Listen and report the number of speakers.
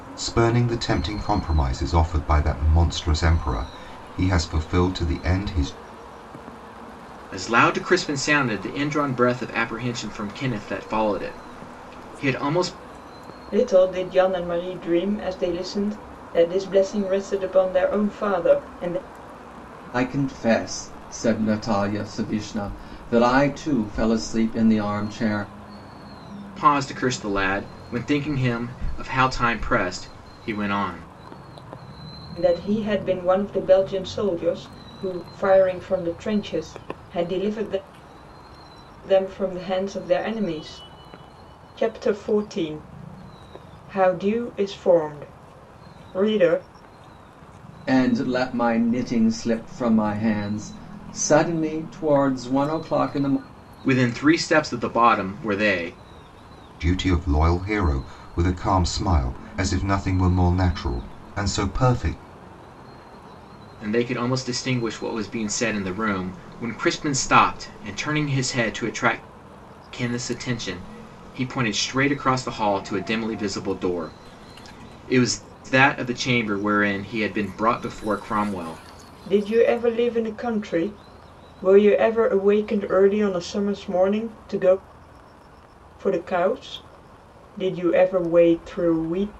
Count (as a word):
four